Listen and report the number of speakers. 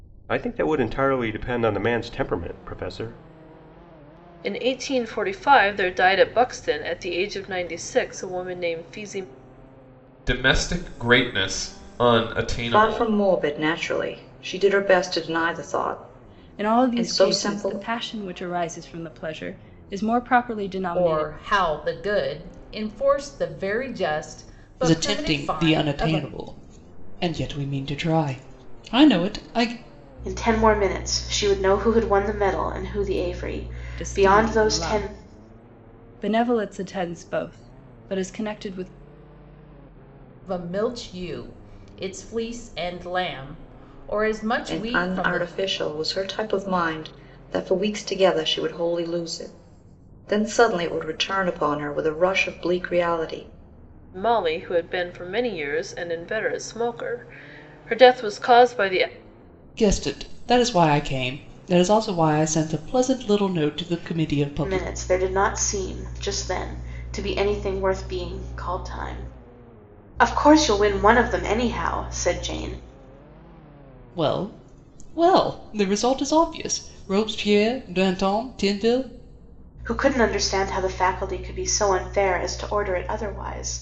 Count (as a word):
eight